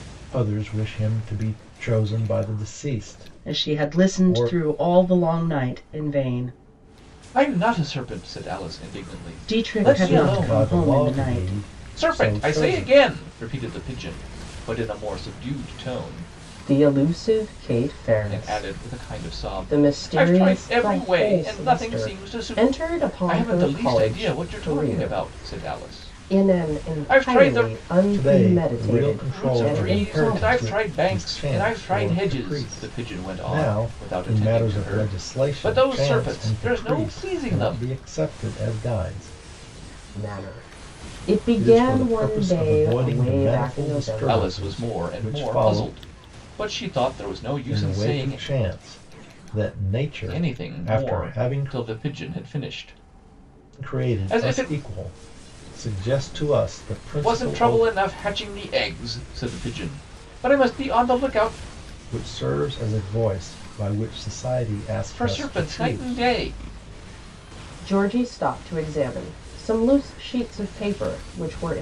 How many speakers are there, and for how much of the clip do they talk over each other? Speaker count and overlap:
three, about 43%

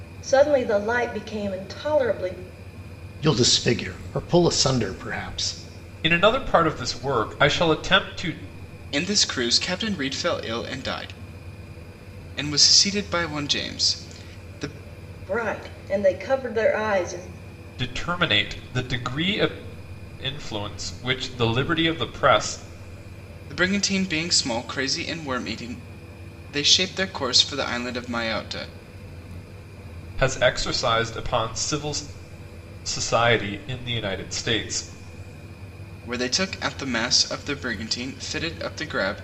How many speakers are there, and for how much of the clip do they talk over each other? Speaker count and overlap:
four, no overlap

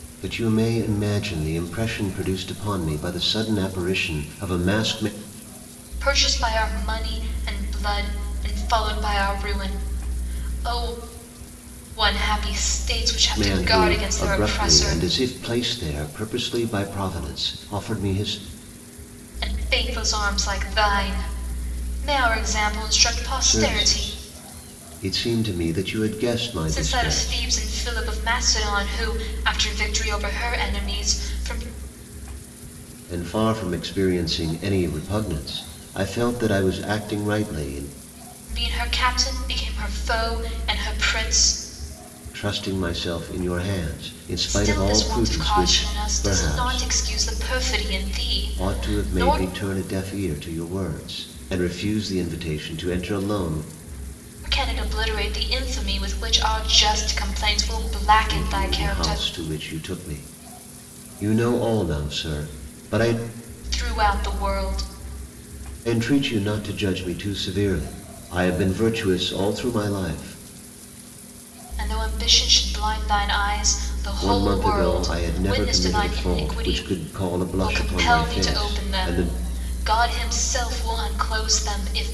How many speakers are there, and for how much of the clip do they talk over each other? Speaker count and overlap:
two, about 14%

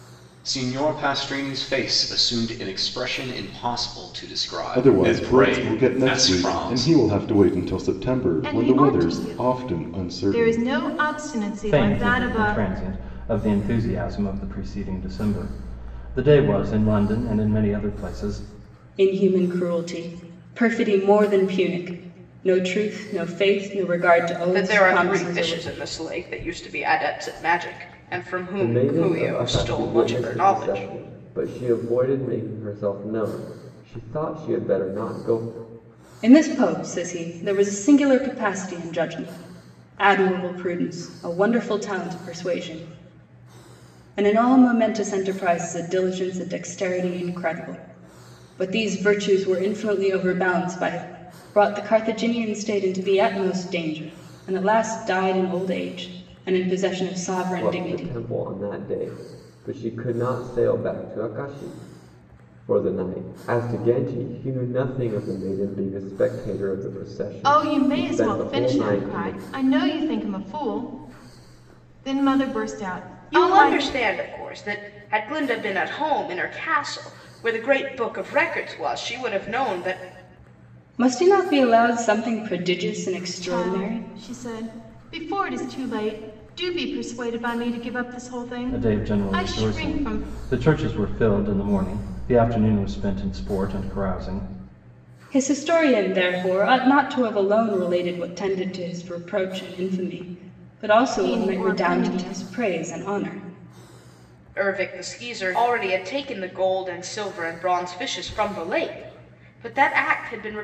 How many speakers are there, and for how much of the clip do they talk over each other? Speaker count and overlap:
seven, about 14%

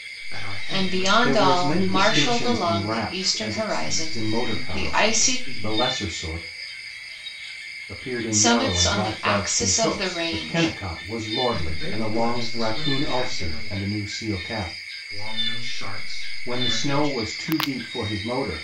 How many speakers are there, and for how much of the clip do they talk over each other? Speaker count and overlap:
three, about 55%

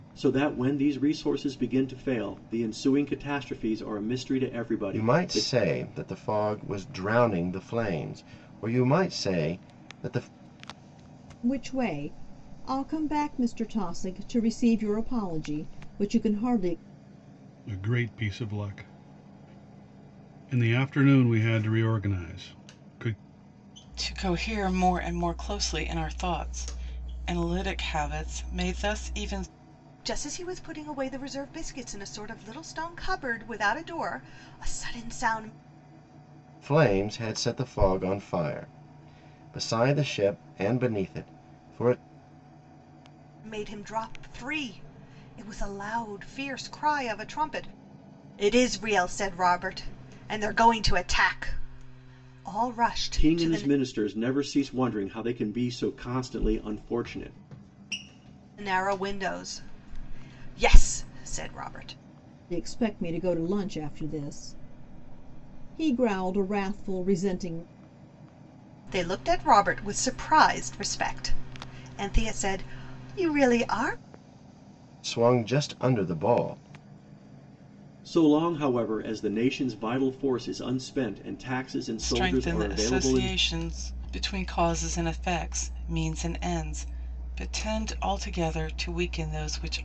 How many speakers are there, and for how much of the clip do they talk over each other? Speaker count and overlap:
six, about 3%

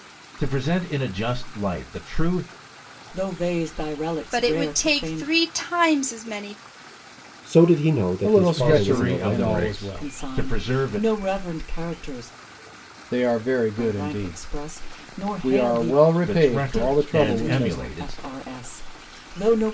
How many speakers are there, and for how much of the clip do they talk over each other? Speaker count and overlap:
five, about 37%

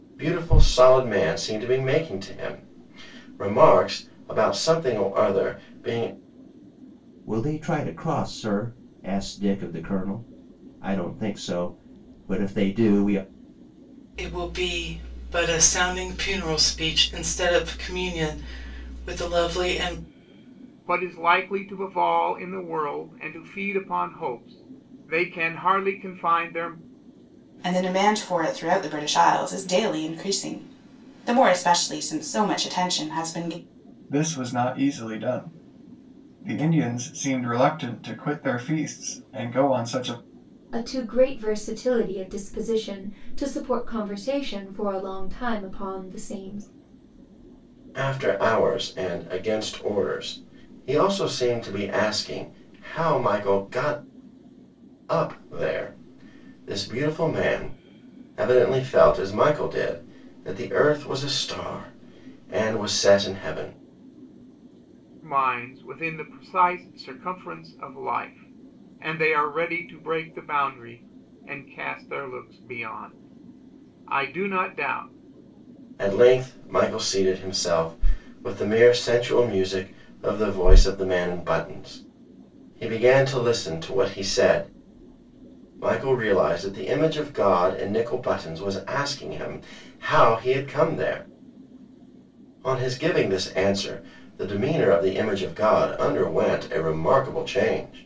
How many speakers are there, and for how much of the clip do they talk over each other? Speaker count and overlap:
seven, no overlap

